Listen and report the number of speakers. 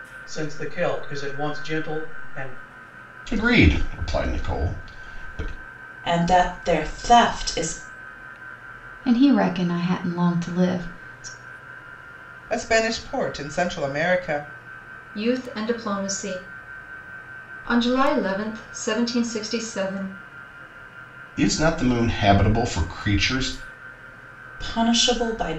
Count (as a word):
six